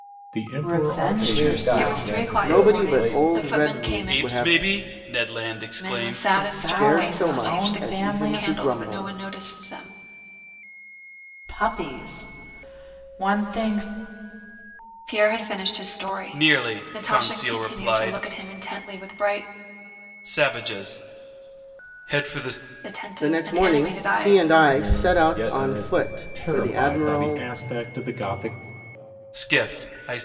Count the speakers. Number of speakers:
6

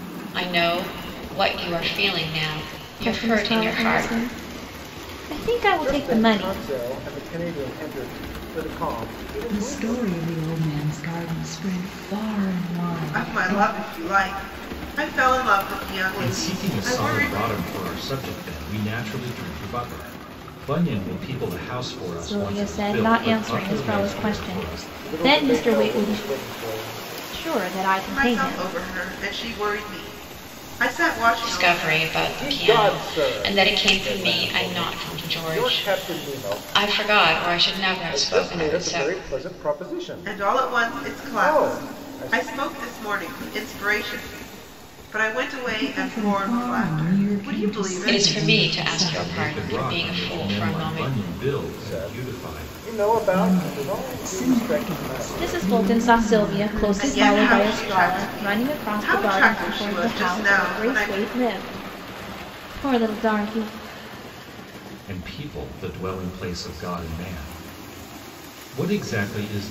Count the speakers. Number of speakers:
6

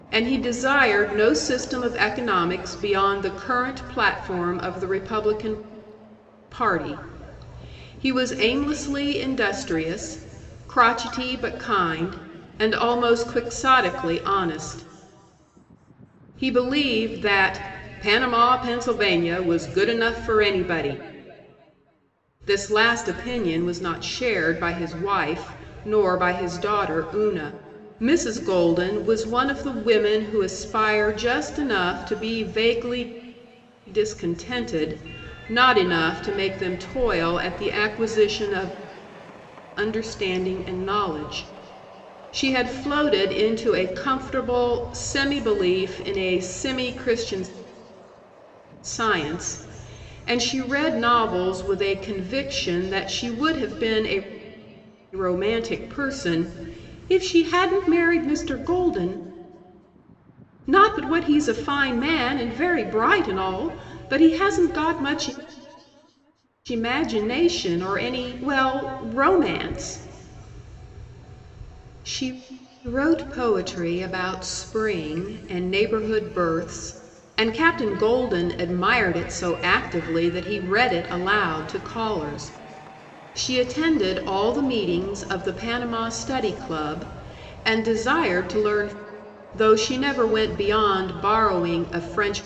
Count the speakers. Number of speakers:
1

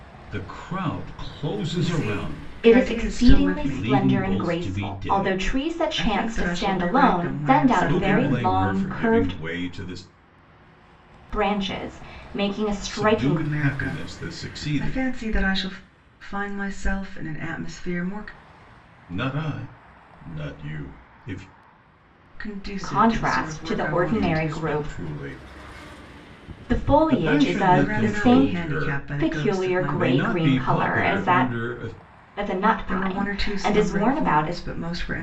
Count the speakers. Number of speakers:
3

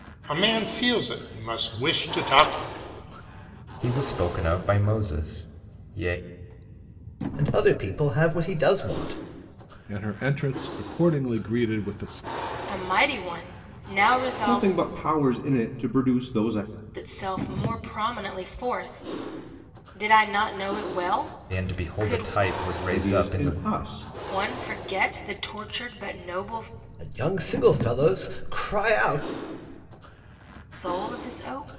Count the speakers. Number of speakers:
6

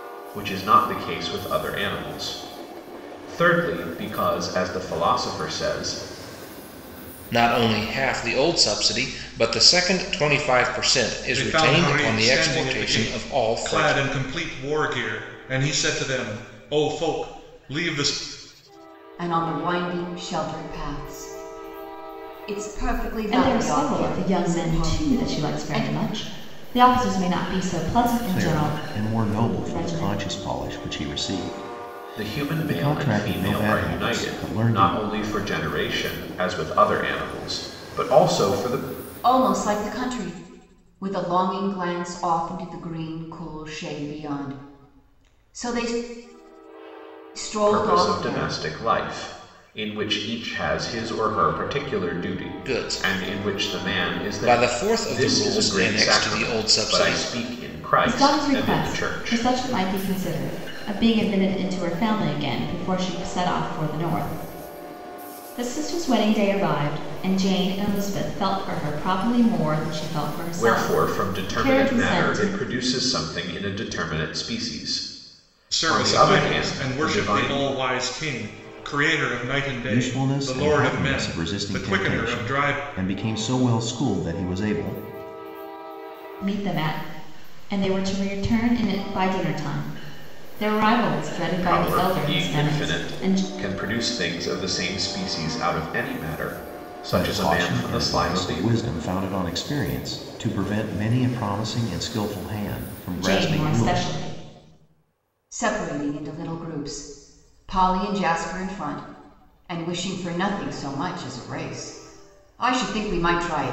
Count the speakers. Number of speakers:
6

